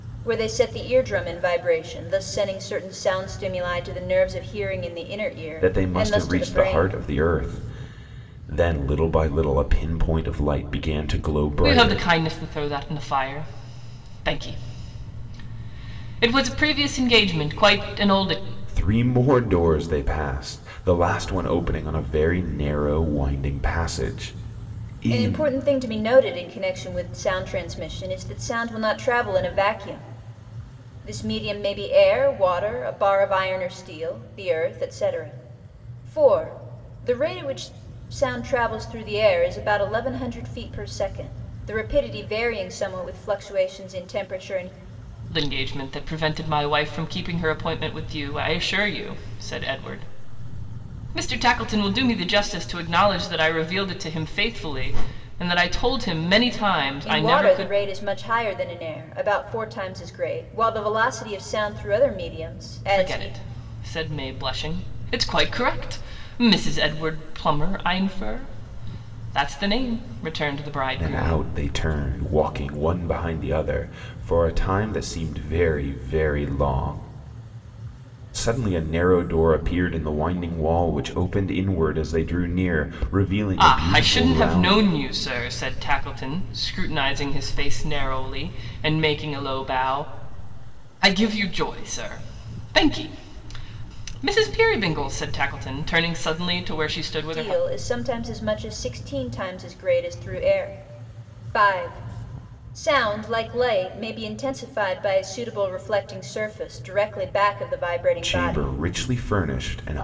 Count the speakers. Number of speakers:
3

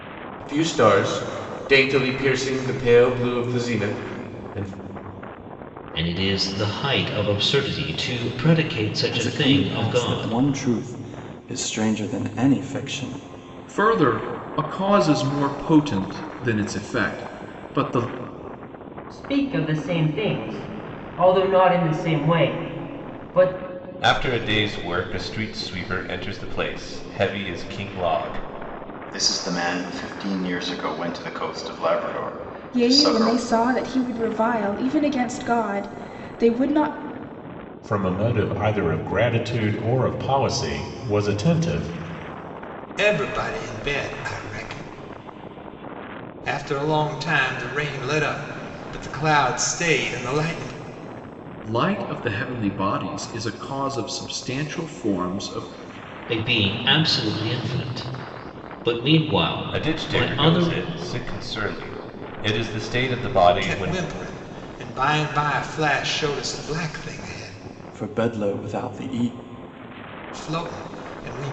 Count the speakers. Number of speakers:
10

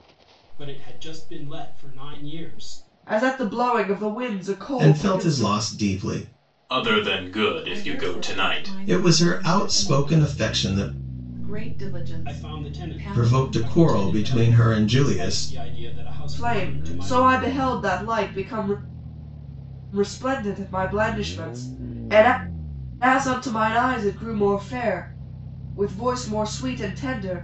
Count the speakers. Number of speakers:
5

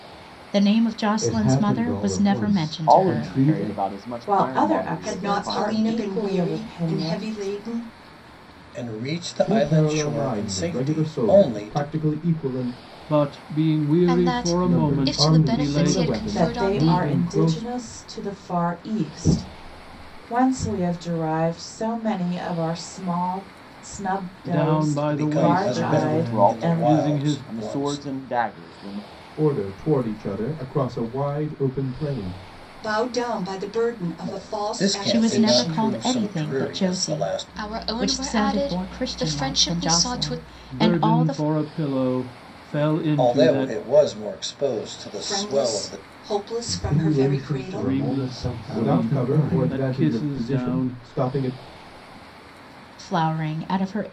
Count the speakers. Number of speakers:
9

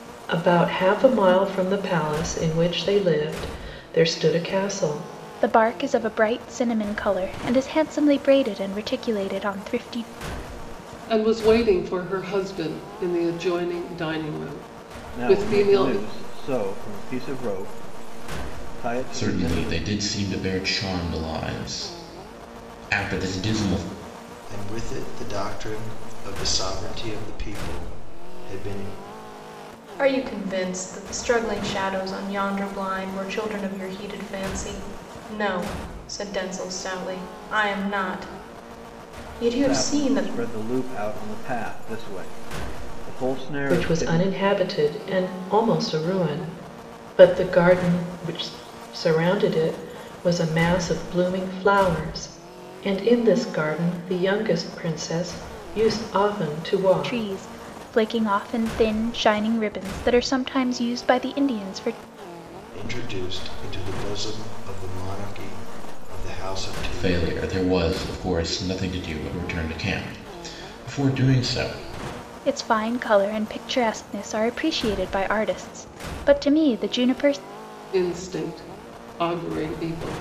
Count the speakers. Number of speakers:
7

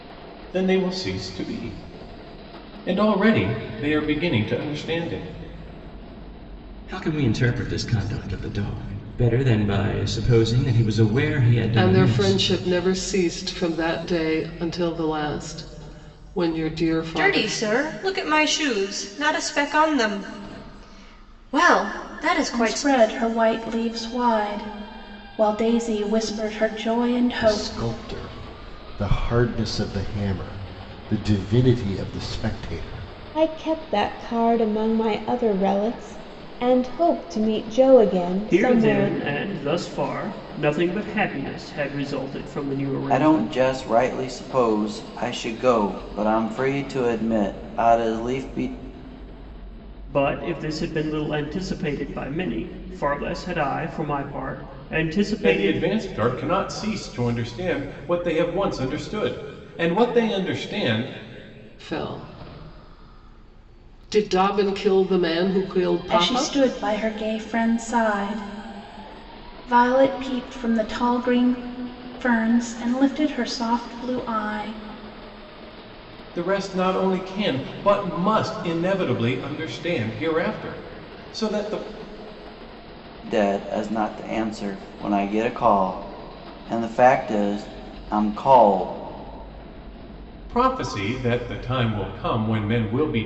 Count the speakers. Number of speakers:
9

